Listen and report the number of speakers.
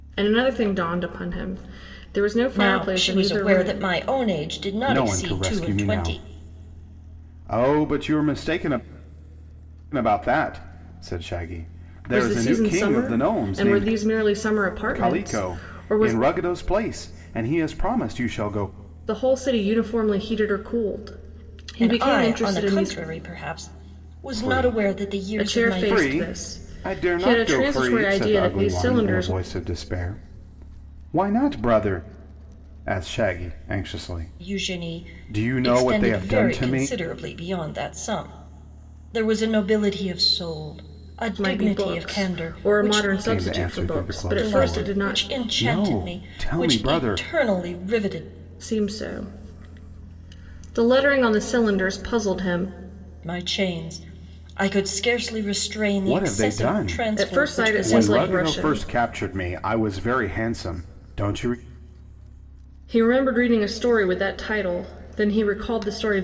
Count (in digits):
3